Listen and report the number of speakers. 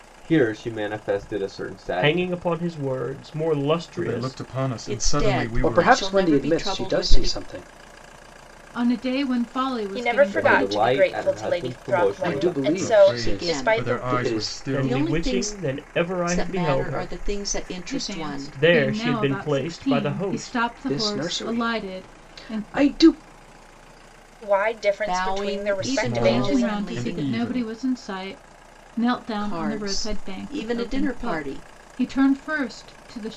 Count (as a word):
seven